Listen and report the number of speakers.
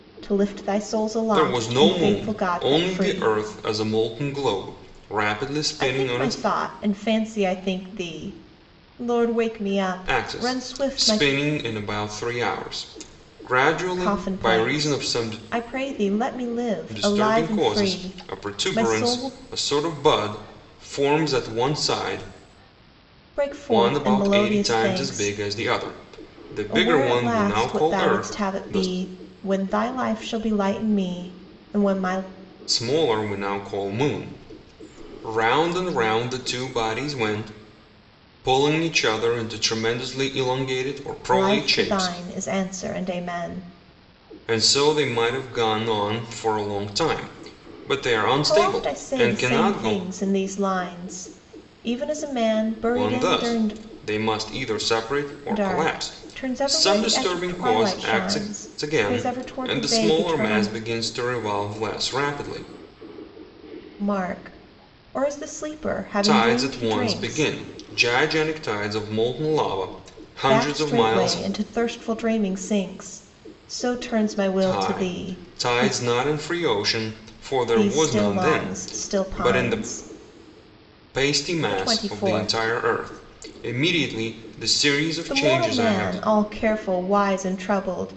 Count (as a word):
two